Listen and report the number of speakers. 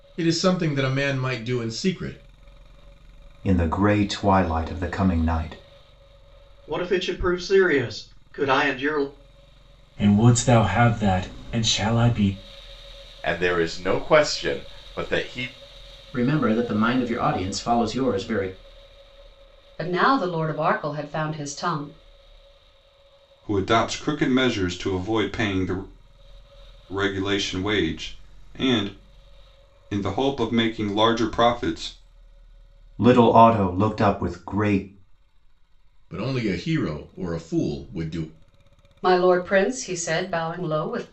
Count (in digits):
8